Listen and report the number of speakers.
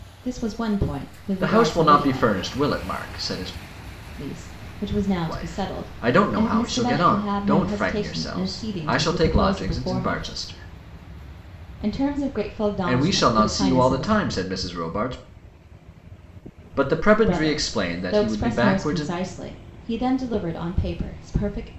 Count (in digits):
2